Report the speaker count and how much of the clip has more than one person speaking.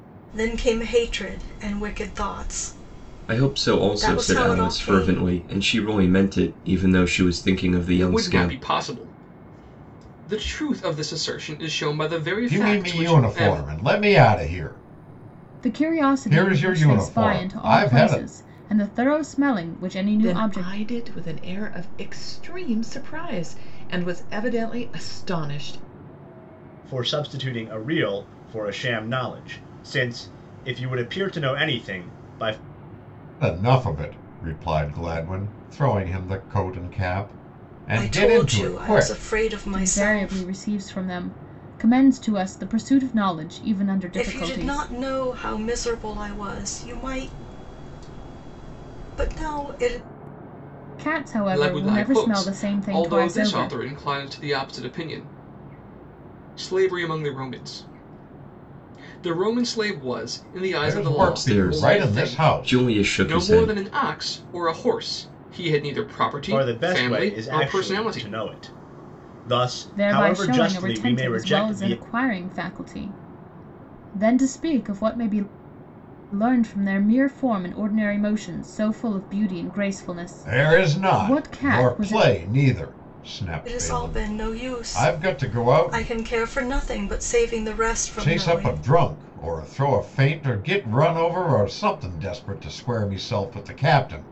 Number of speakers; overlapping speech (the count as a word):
seven, about 25%